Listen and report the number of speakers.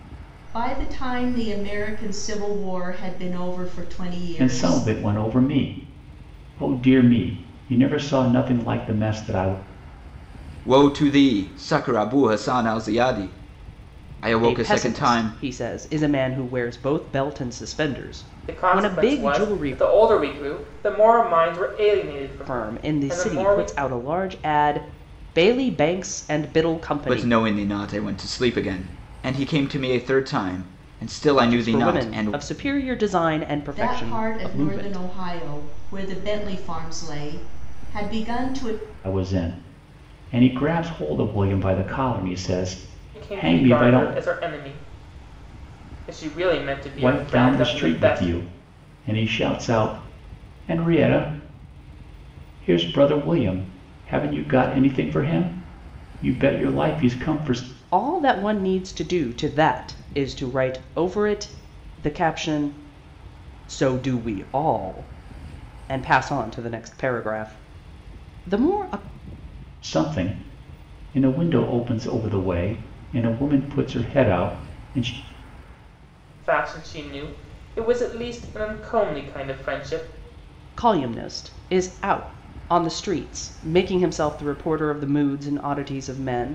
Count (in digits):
5